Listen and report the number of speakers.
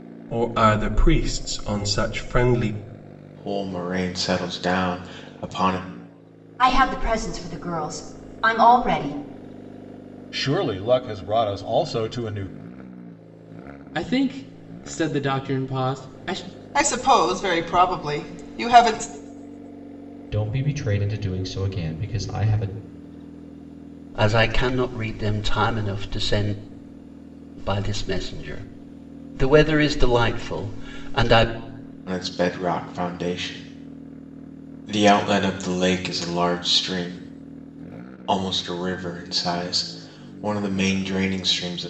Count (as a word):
eight